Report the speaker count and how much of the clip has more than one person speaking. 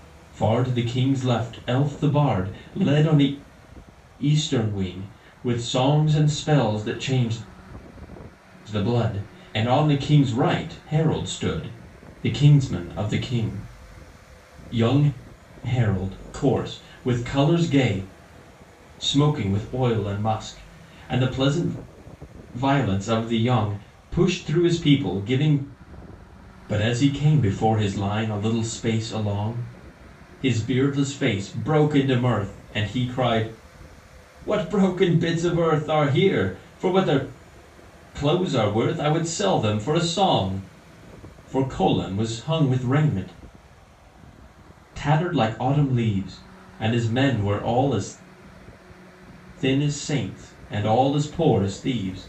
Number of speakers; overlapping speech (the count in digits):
1, no overlap